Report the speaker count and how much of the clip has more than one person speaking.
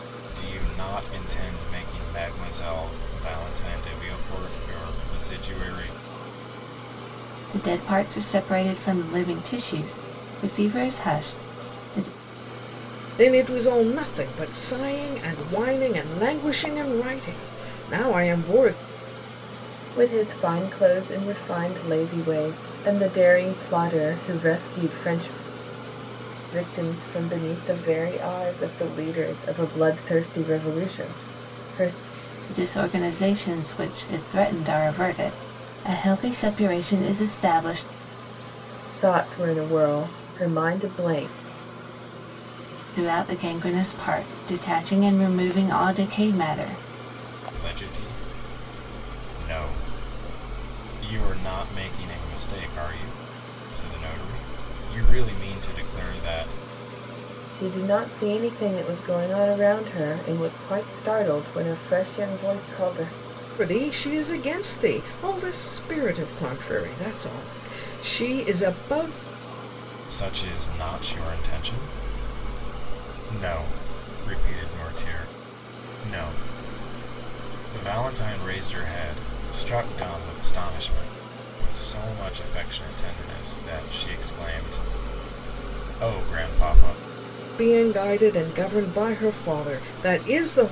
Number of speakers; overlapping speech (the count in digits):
4, no overlap